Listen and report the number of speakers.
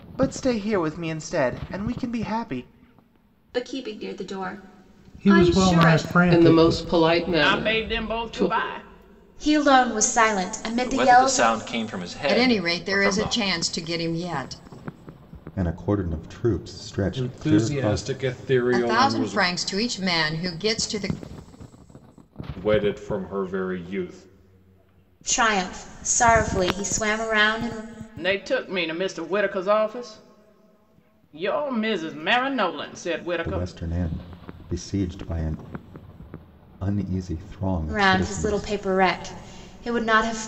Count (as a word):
ten